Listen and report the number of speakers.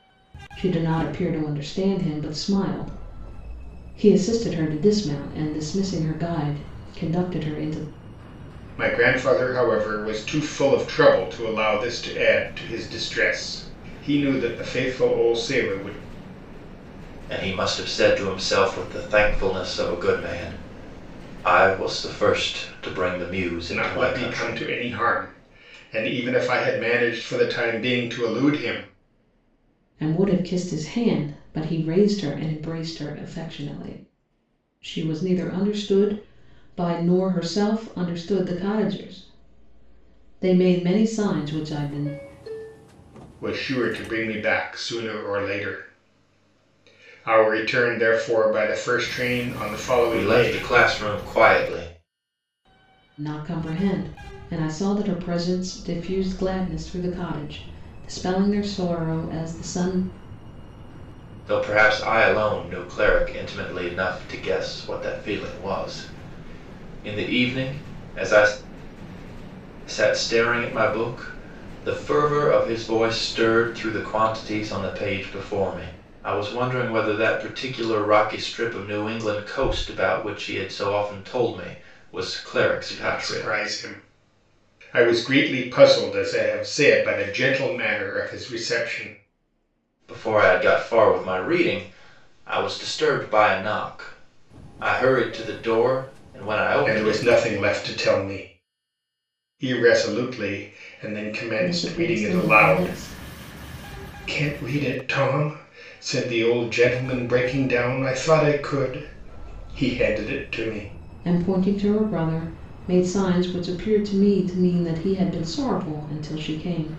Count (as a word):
three